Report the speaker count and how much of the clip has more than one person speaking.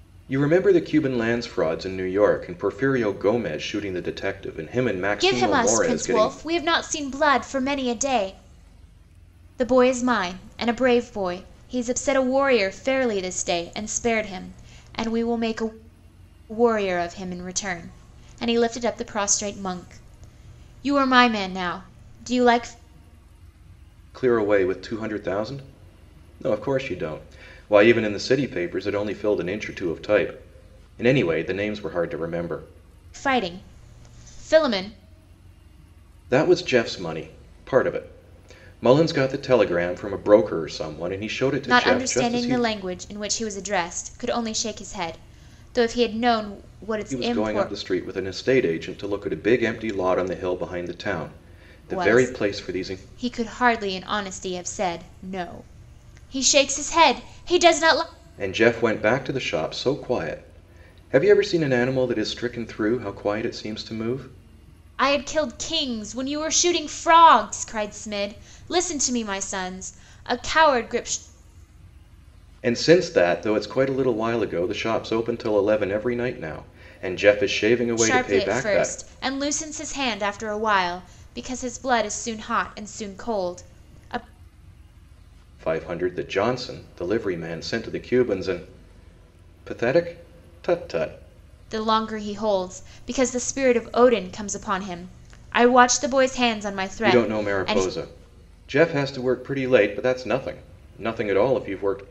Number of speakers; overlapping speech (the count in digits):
2, about 6%